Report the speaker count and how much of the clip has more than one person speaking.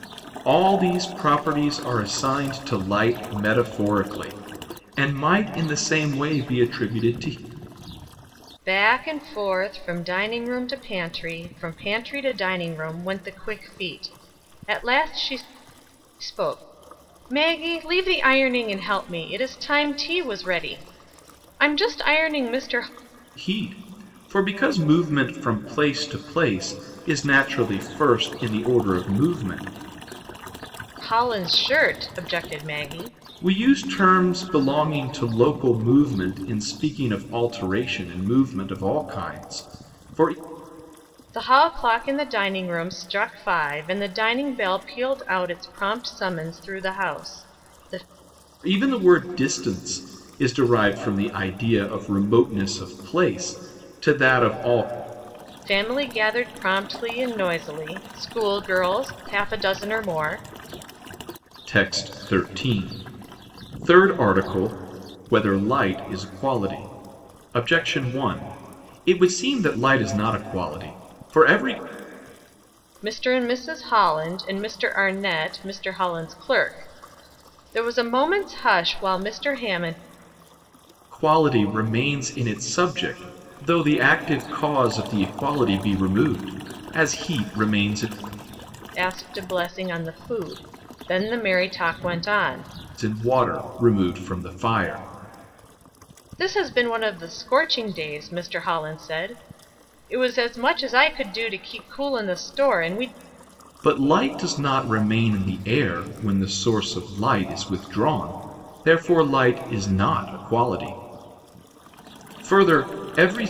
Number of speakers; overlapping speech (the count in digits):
2, no overlap